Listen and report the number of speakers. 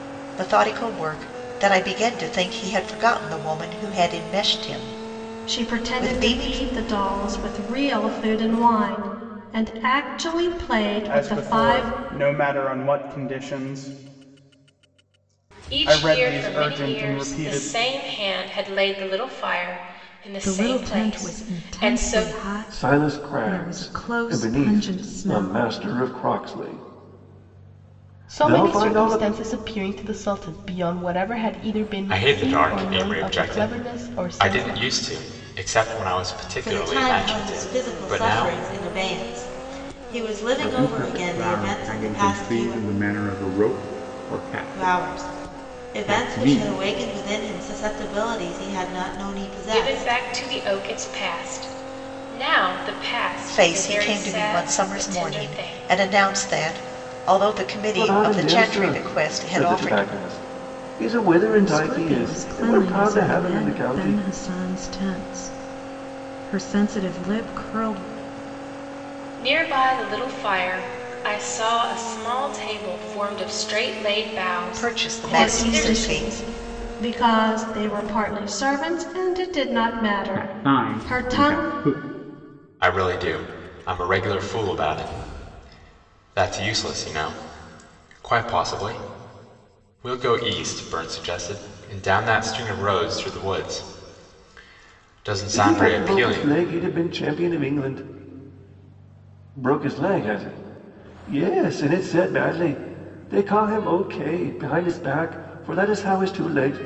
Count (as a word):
ten